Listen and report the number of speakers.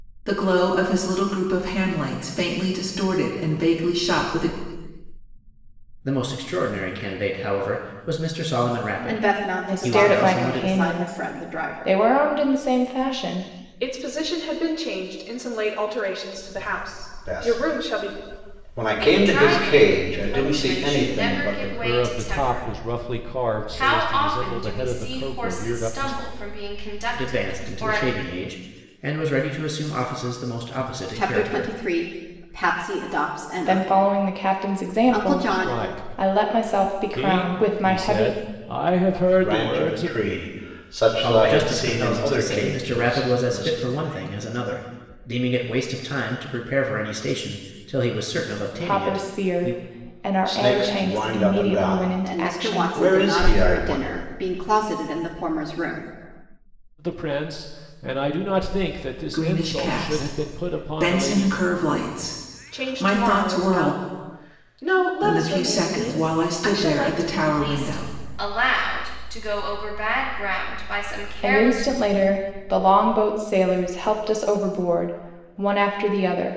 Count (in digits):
8